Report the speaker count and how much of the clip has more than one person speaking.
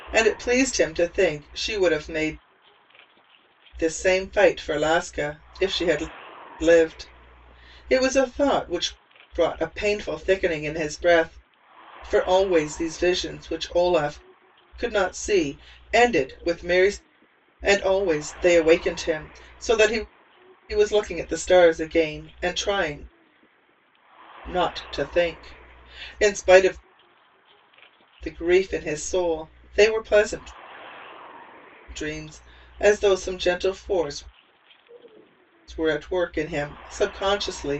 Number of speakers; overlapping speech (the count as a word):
one, no overlap